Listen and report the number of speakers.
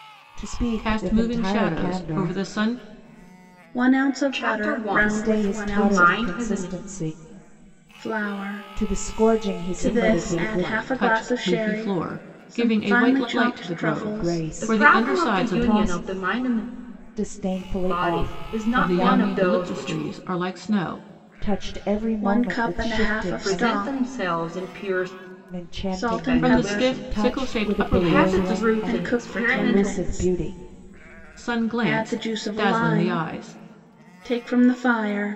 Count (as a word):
four